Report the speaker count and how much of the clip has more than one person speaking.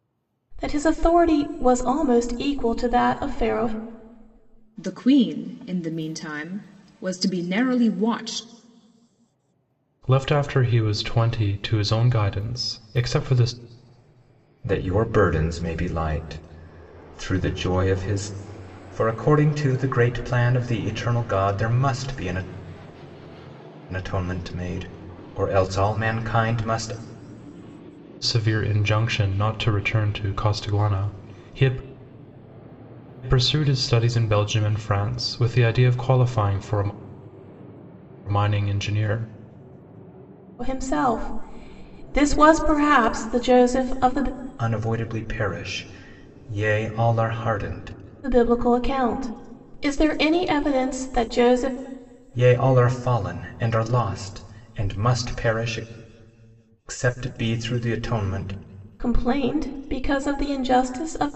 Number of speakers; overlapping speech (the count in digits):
4, no overlap